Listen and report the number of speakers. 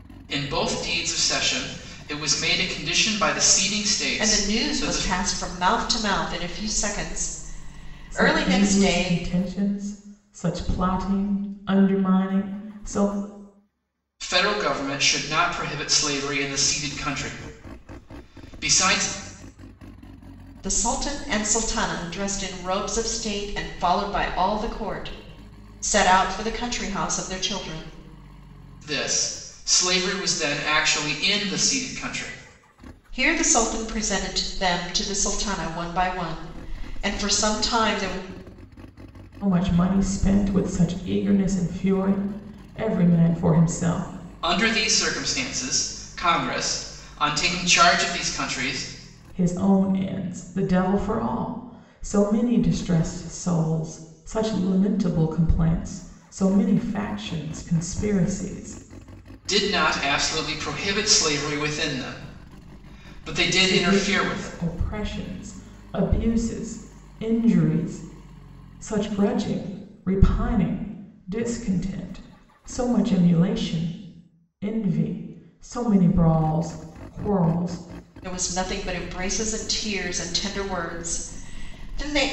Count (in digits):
3